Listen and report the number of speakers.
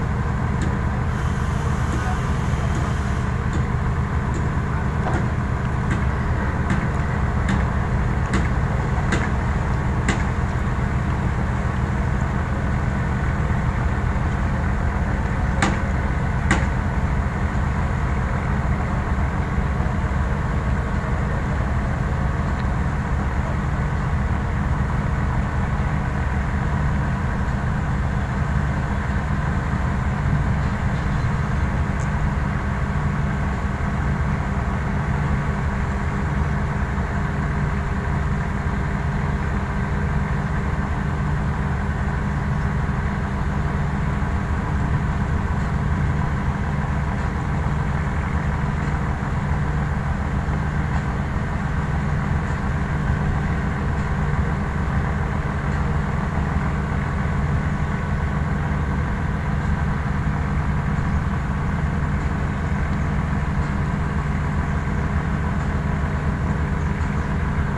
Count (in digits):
0